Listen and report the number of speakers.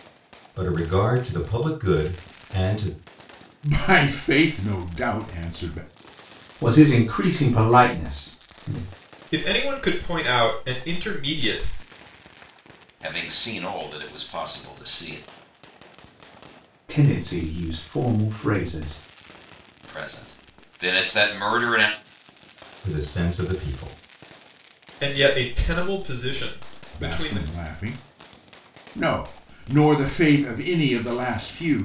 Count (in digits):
5